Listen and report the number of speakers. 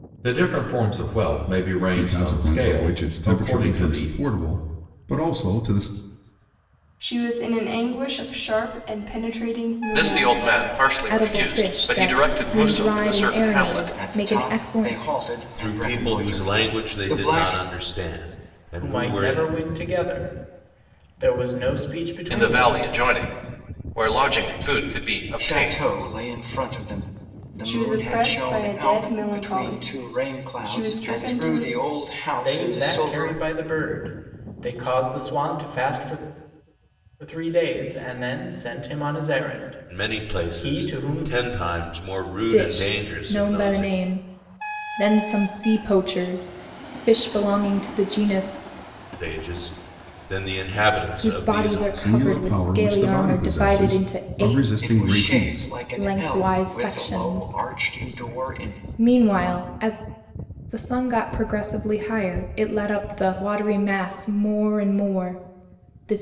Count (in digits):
8